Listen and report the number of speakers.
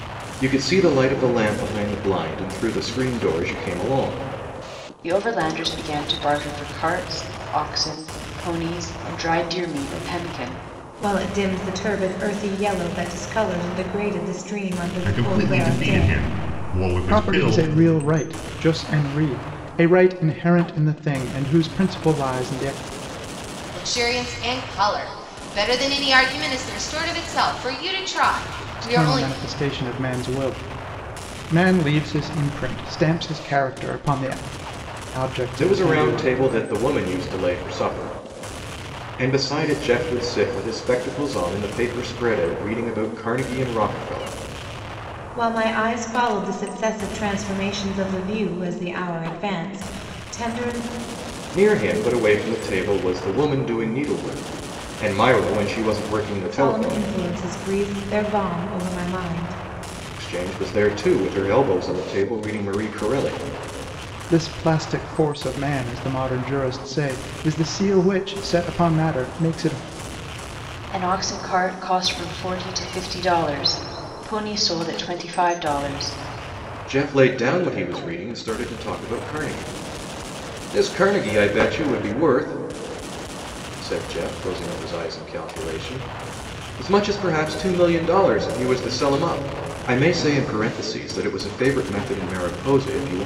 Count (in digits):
6